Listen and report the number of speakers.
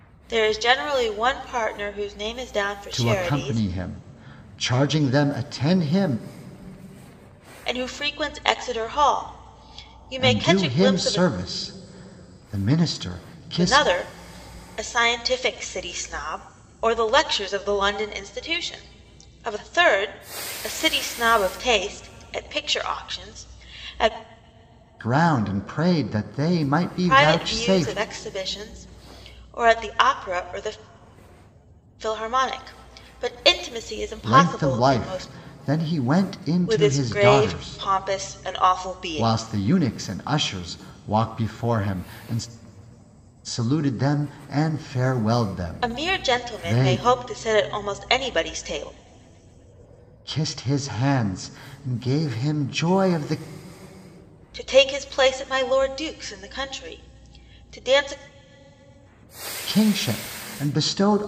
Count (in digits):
2